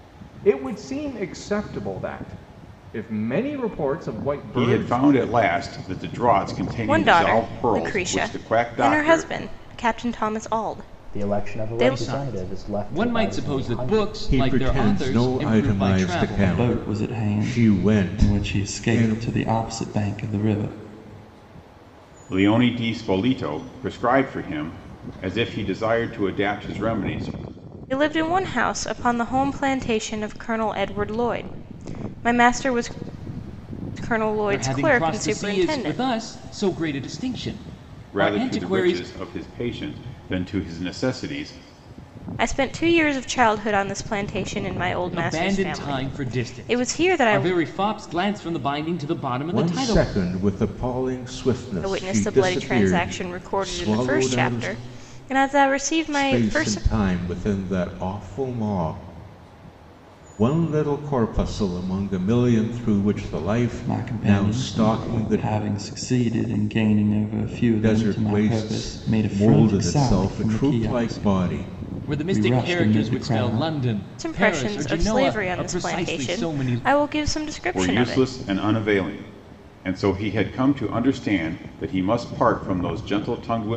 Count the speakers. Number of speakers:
7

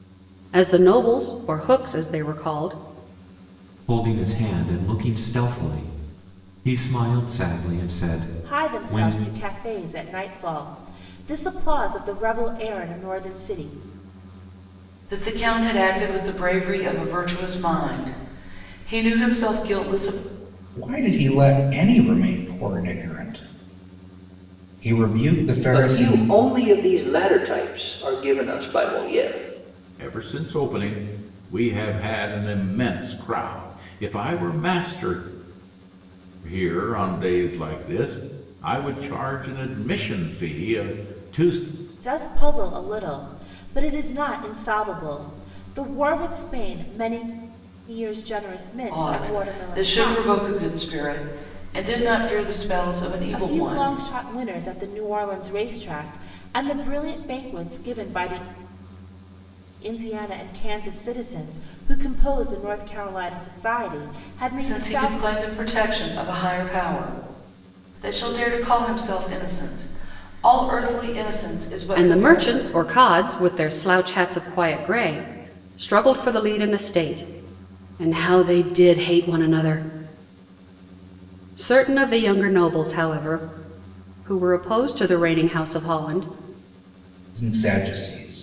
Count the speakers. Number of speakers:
7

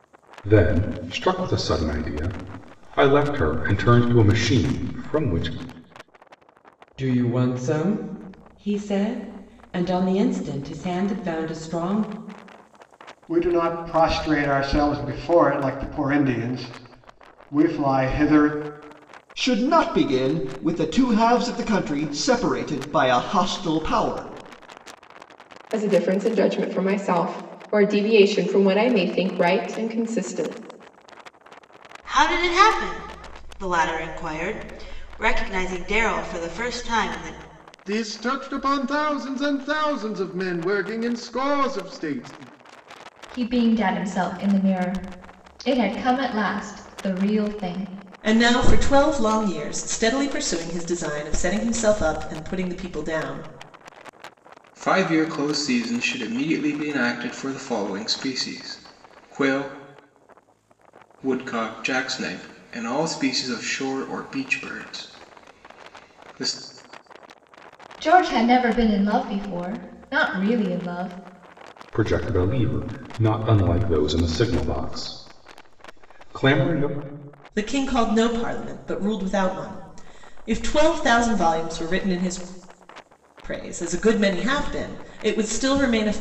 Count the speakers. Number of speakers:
10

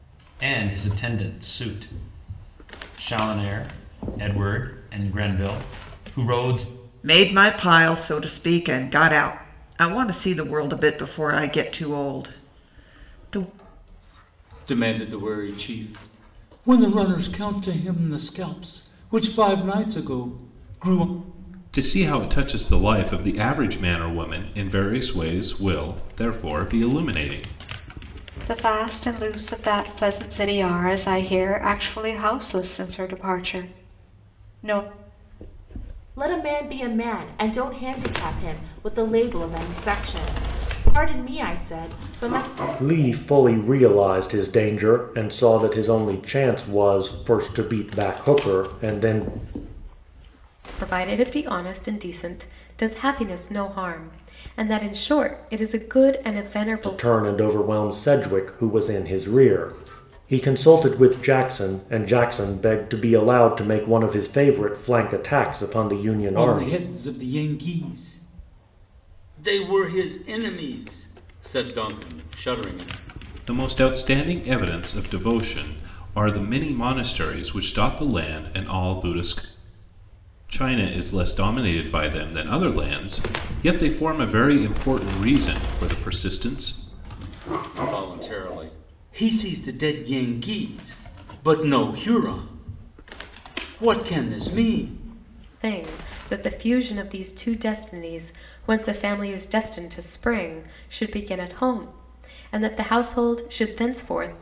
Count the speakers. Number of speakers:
8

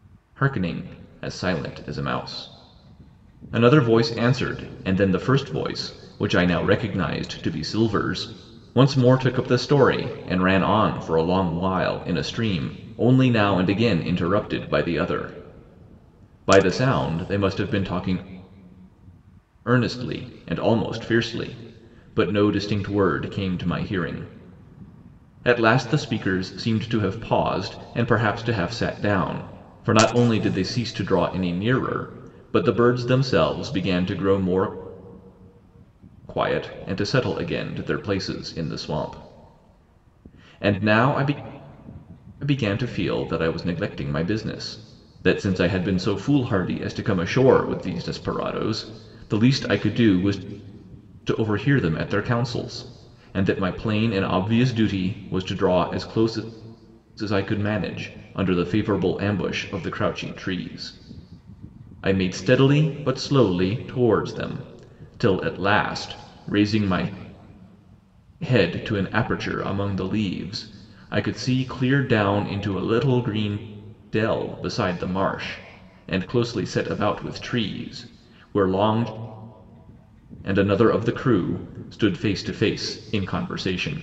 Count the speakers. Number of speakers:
1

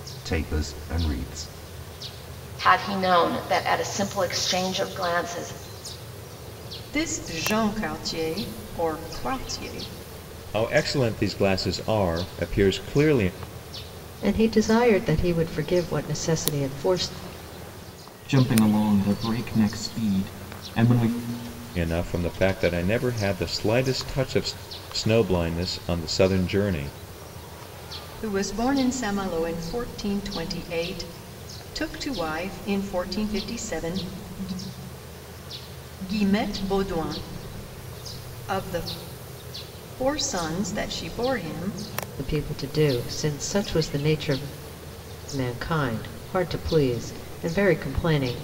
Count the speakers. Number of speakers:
6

